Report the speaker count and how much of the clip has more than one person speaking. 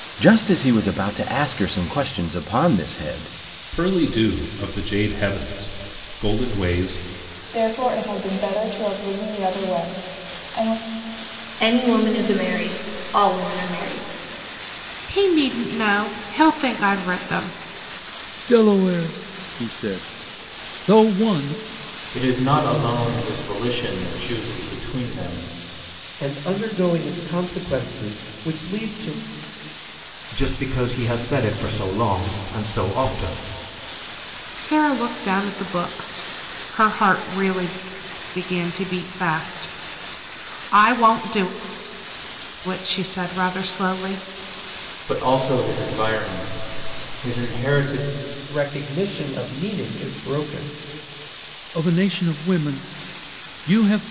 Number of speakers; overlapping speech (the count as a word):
nine, no overlap